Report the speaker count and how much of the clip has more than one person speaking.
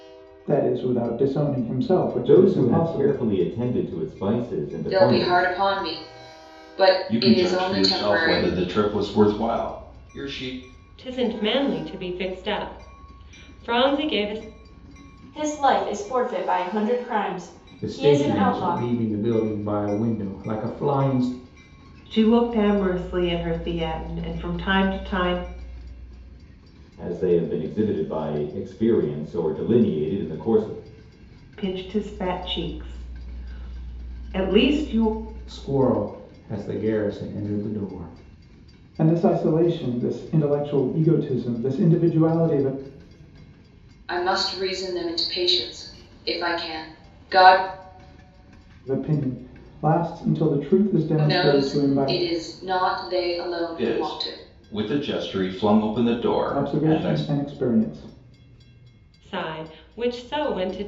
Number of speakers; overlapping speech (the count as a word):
eight, about 11%